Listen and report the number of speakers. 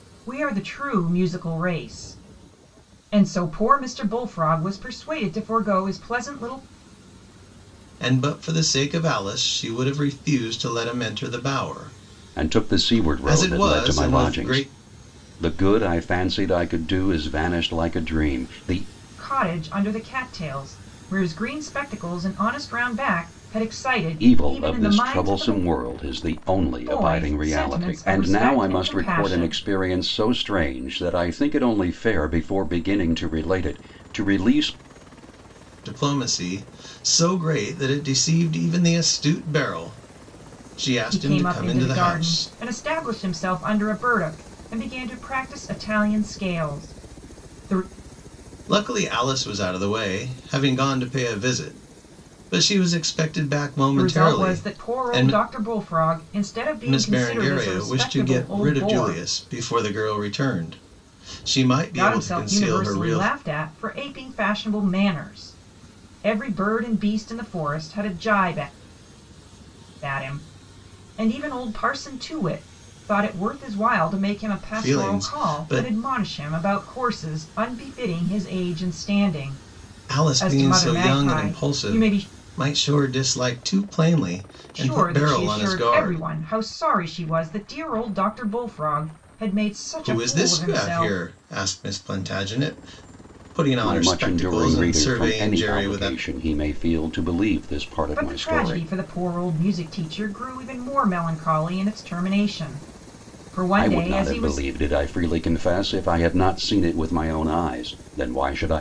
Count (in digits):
3